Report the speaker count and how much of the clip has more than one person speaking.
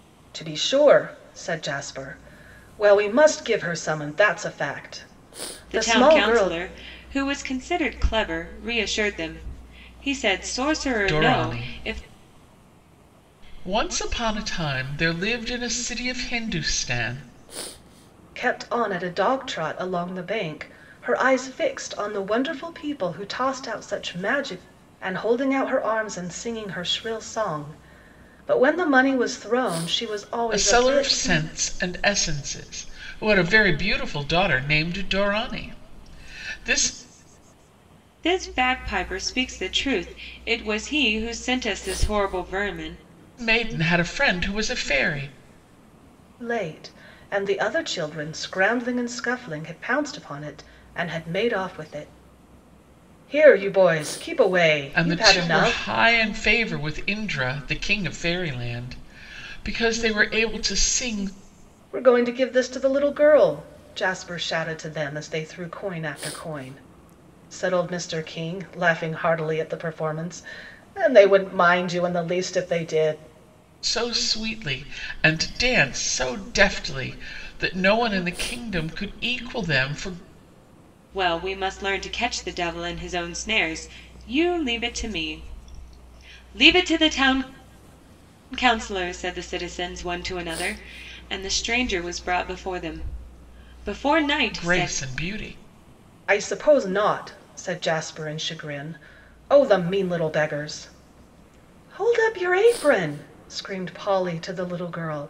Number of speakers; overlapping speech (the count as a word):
three, about 4%